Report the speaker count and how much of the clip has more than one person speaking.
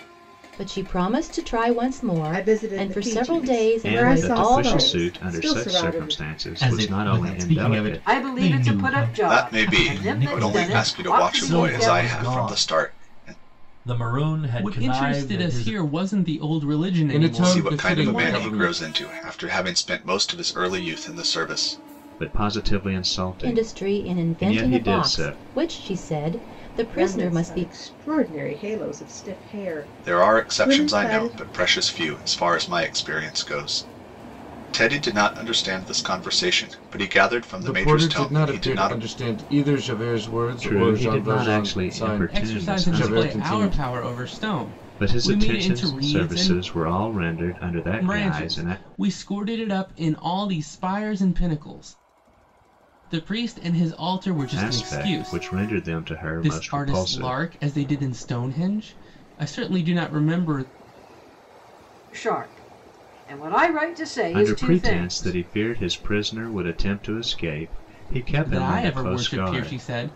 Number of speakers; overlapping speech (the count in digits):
9, about 42%